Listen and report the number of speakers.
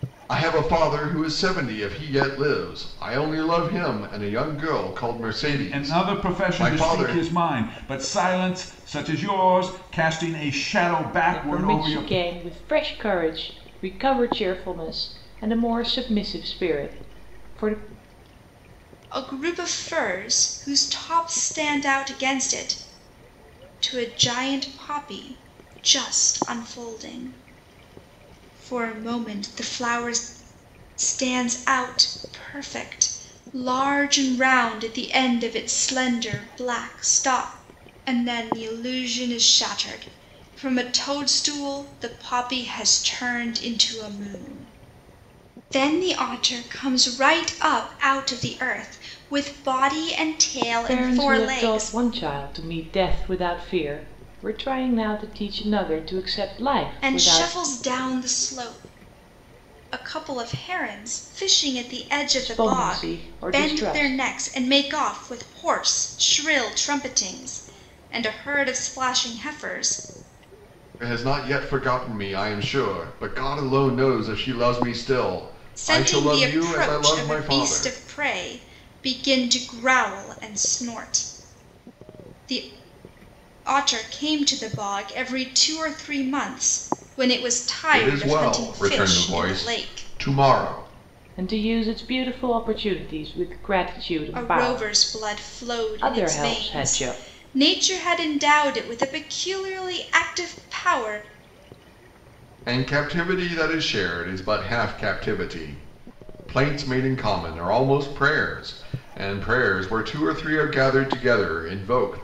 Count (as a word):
four